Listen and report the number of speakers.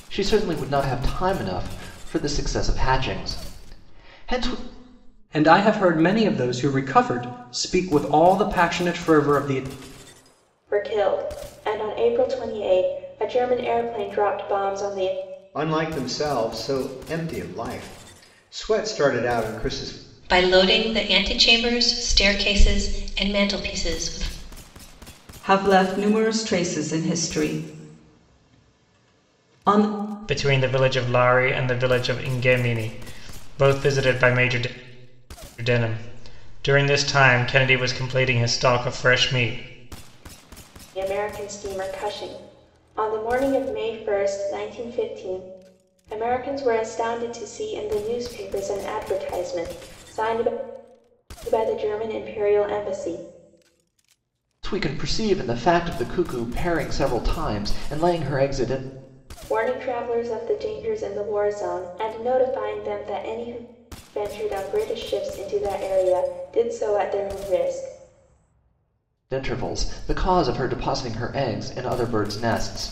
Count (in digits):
7